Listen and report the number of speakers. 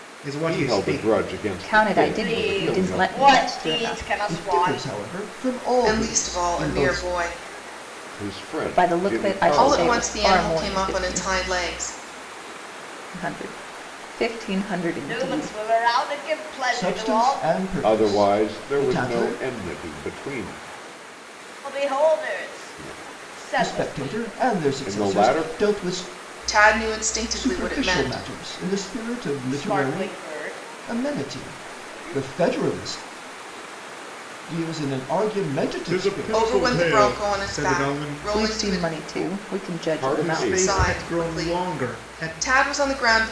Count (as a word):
six